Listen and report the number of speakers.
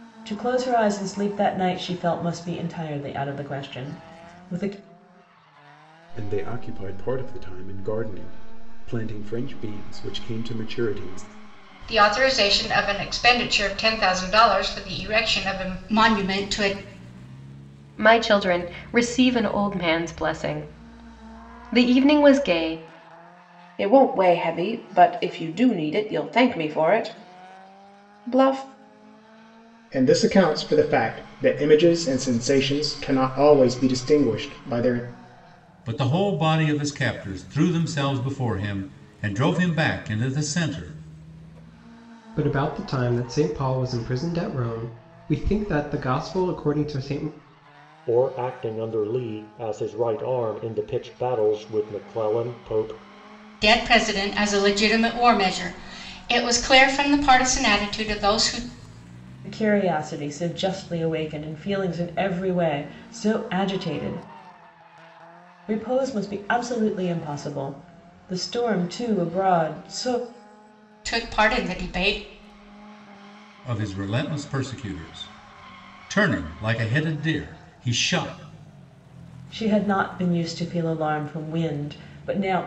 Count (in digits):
9